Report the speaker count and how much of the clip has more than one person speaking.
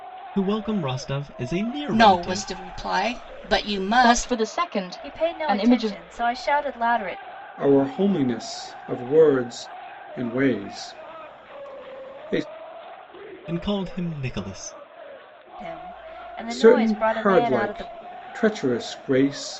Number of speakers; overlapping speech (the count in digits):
5, about 18%